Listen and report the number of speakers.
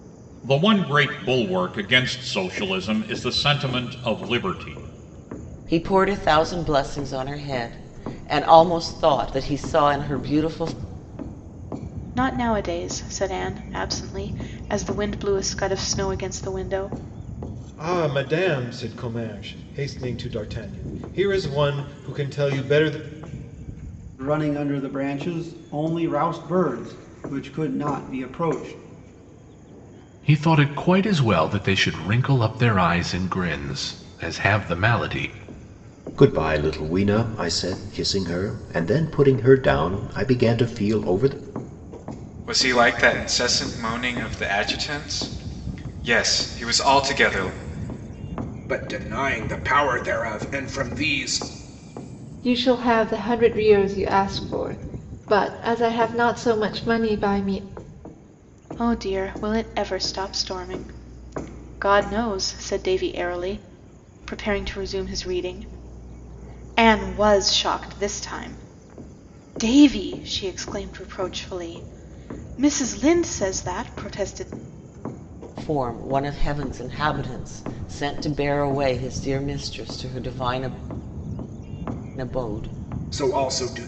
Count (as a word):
ten